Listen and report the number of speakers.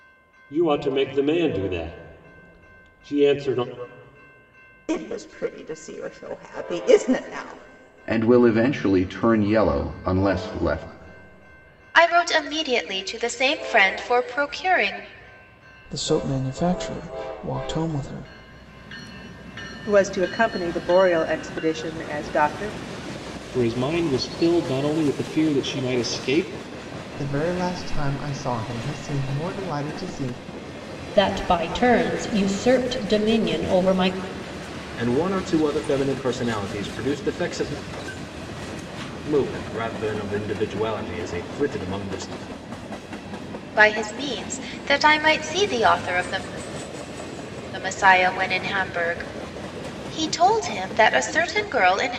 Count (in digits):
10